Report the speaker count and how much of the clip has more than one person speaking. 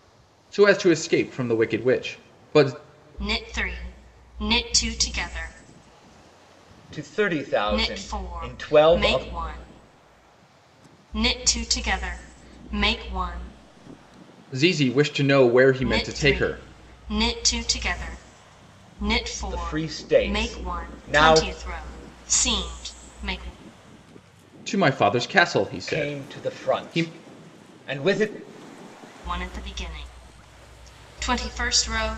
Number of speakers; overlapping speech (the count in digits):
3, about 18%